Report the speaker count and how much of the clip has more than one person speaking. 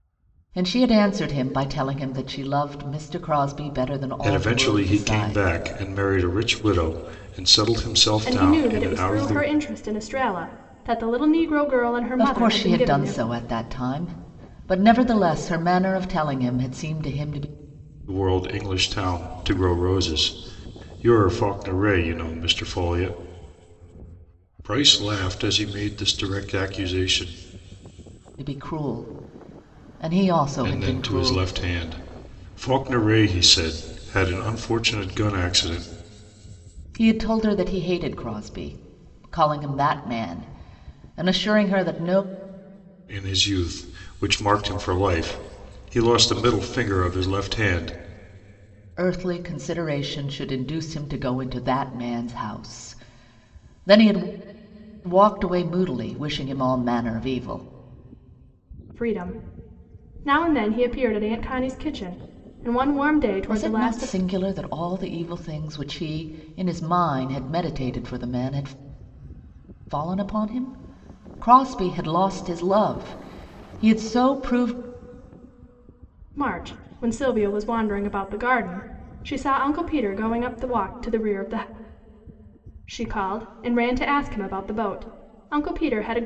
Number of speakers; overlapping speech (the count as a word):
three, about 6%